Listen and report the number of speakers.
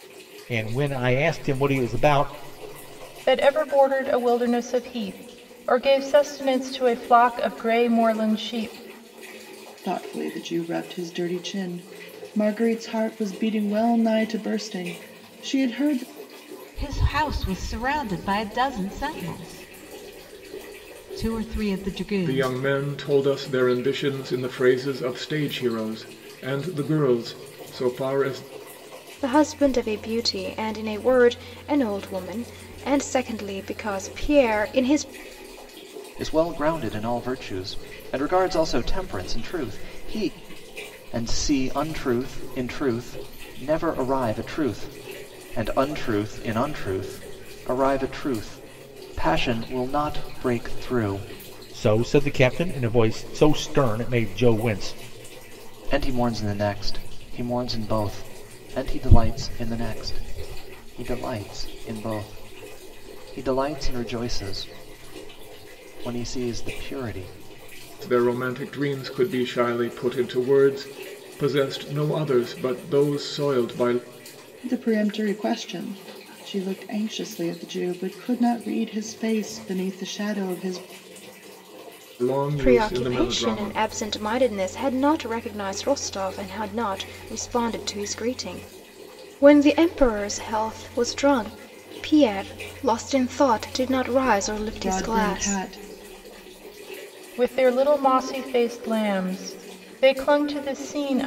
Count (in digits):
7